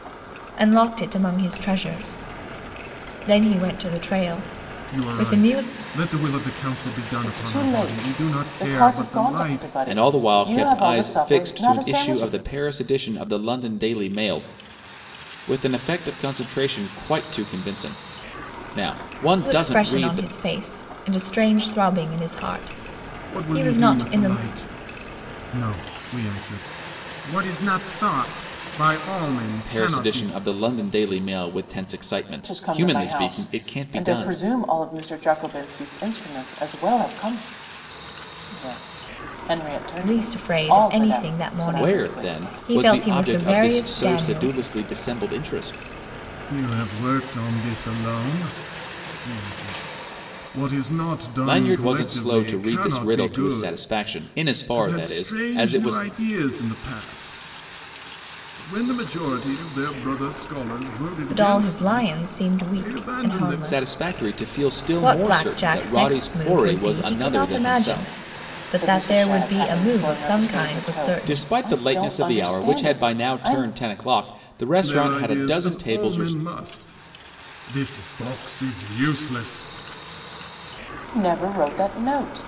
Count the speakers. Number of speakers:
4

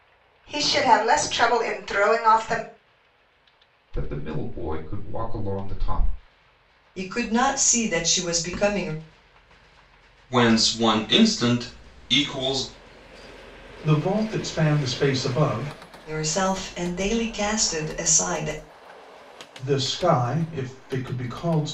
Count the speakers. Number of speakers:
5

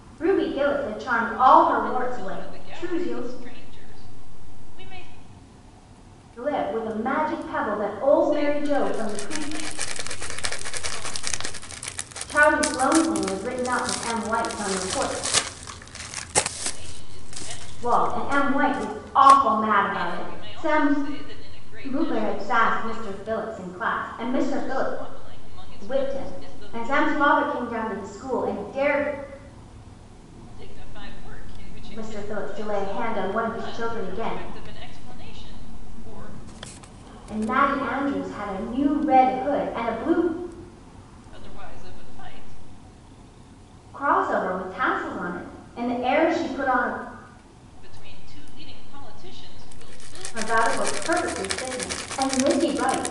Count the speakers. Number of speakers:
2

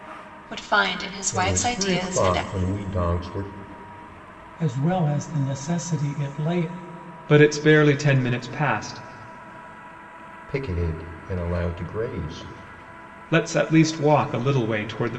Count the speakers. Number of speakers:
4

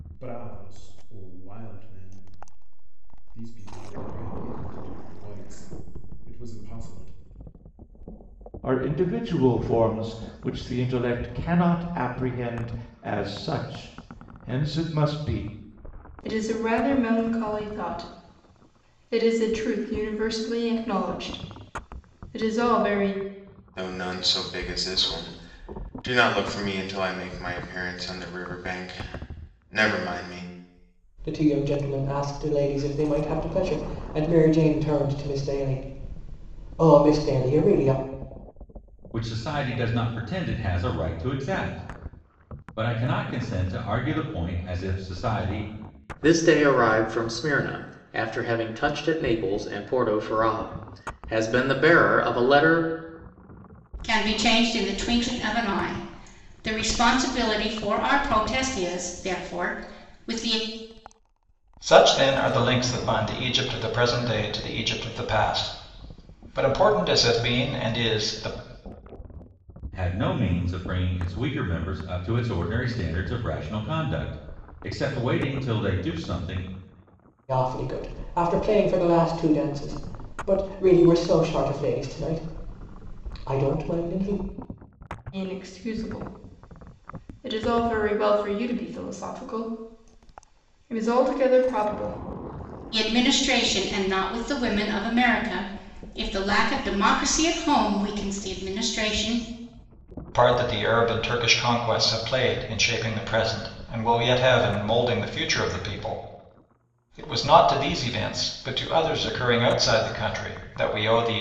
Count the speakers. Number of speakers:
9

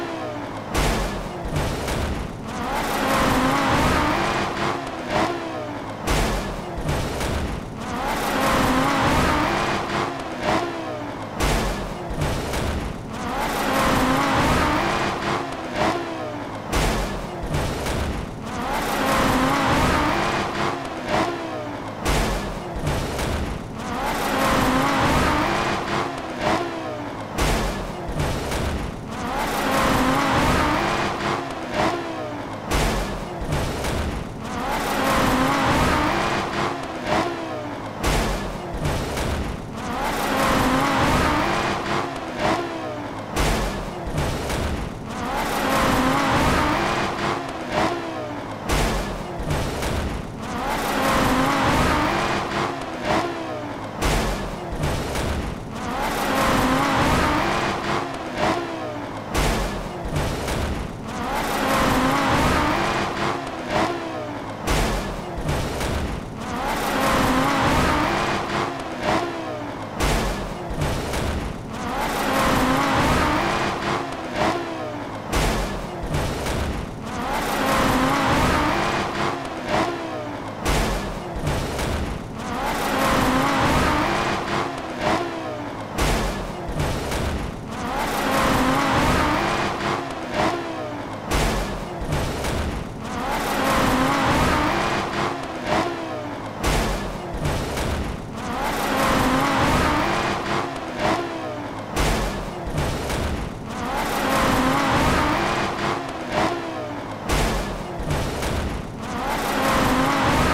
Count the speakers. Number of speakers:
0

